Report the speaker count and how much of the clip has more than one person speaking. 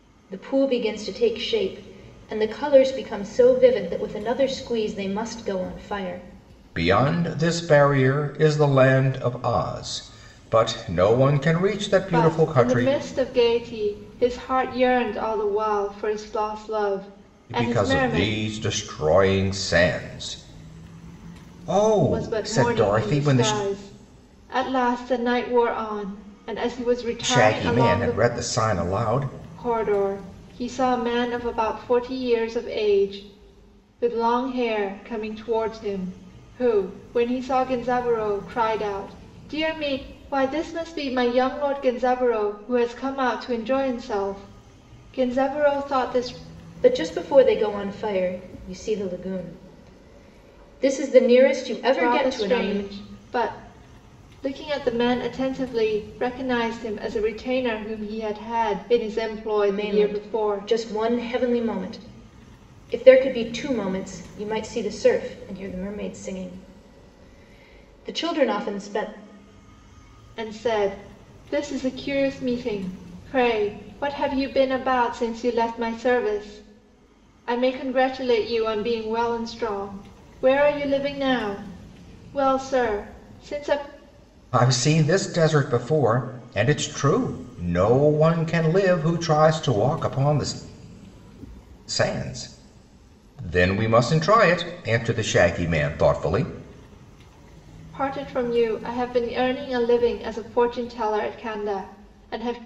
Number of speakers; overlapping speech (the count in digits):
3, about 6%